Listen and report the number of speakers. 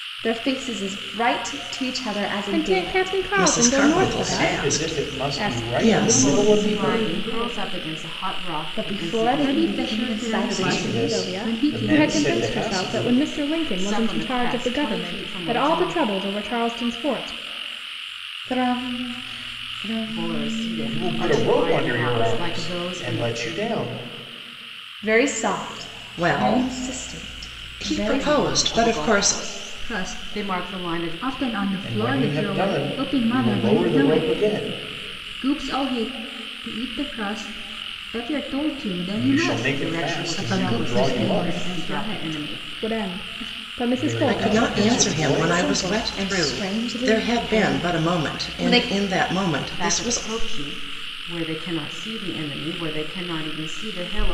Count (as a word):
six